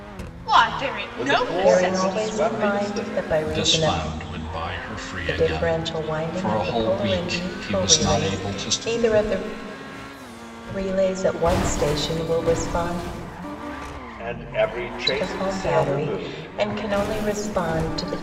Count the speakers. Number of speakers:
four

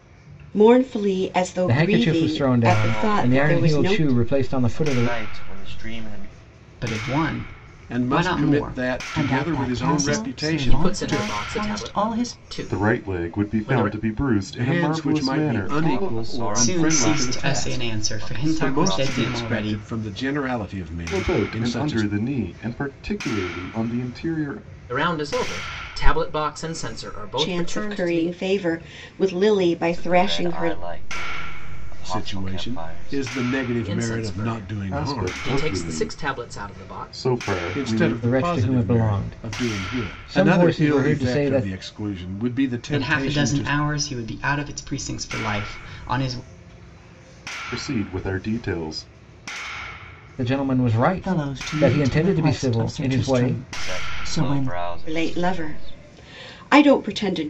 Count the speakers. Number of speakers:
eight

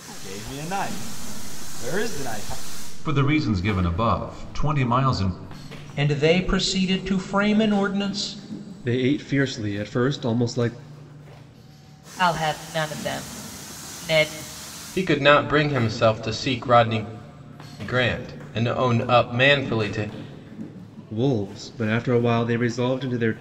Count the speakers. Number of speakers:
six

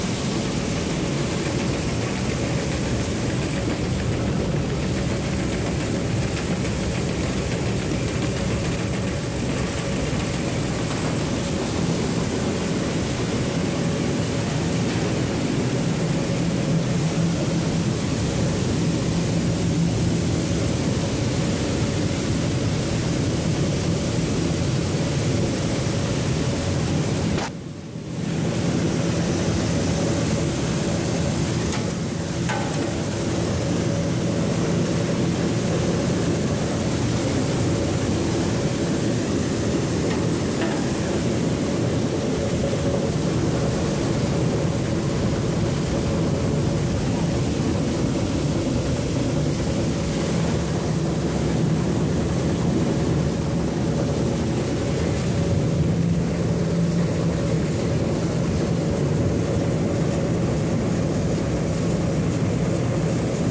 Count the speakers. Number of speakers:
zero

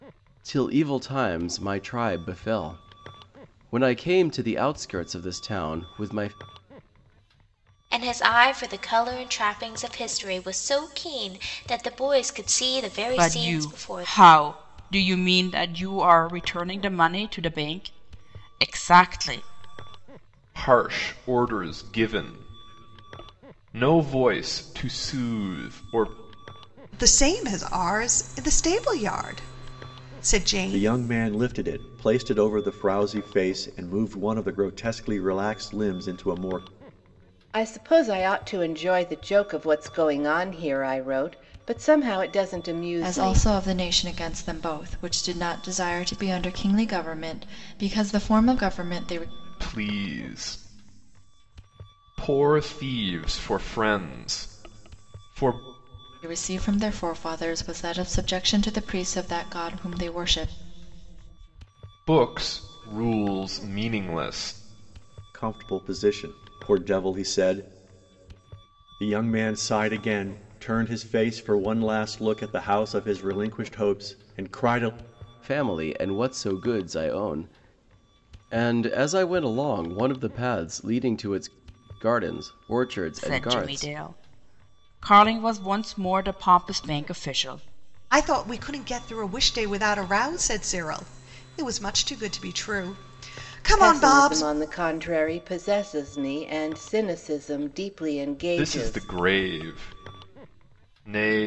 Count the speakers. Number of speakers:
eight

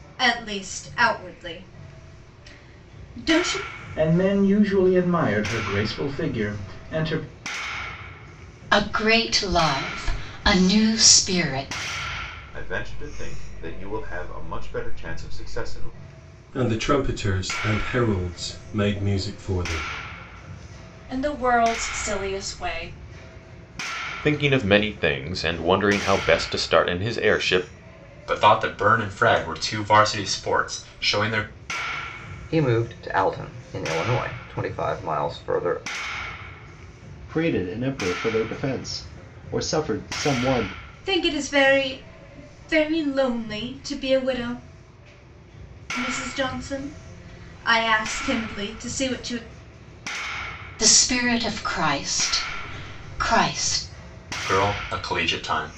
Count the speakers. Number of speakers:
ten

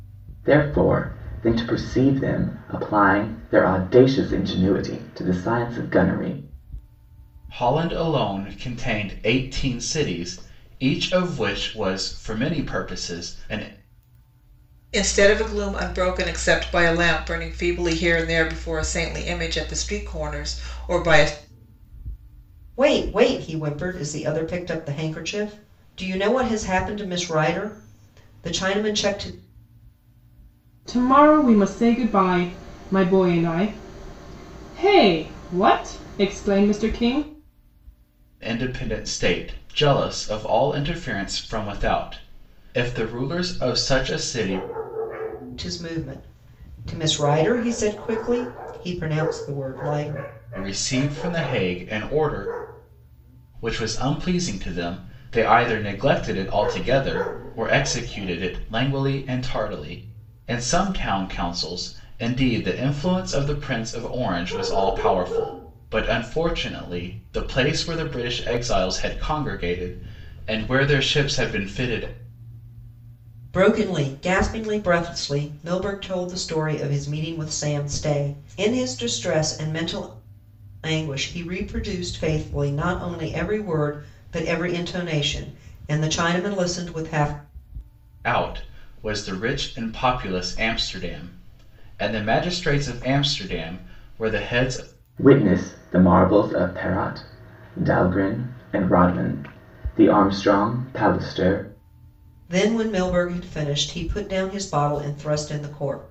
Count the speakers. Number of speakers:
five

